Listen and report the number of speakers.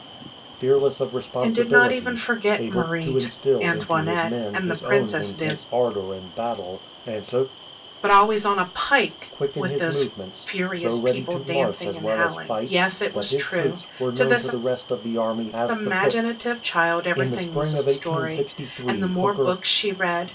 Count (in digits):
2